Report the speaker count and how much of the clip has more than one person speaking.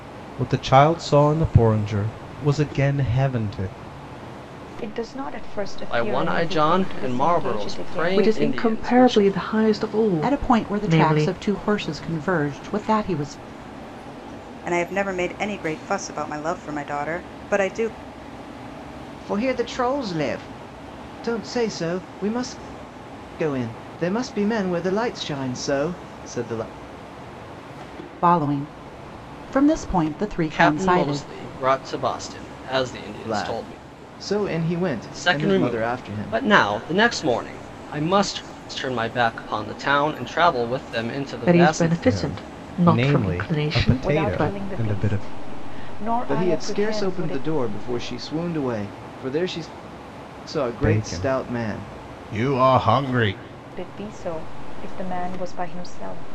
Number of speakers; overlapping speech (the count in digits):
7, about 24%